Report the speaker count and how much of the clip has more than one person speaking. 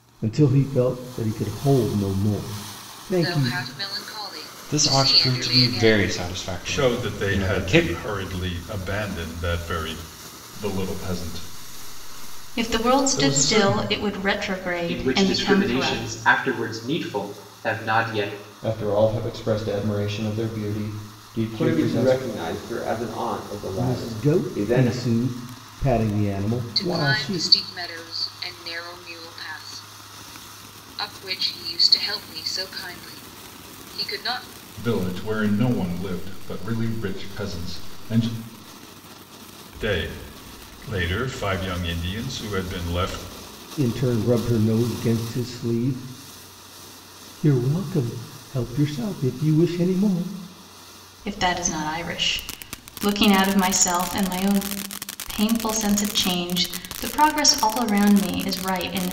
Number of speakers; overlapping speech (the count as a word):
nine, about 14%